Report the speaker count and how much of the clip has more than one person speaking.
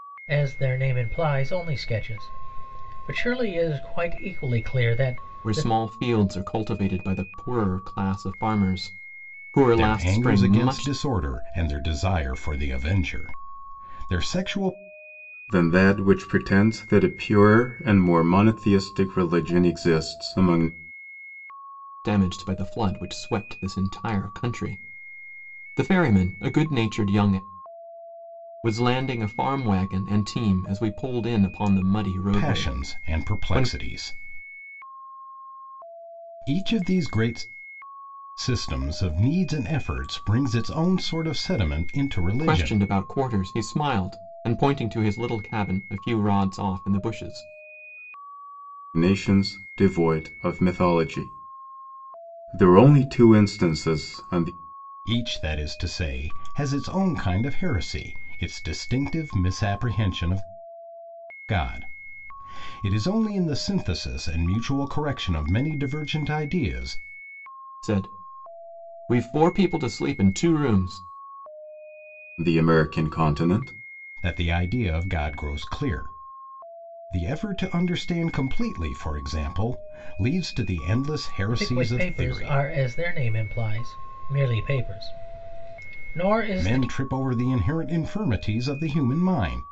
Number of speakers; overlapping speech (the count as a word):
four, about 5%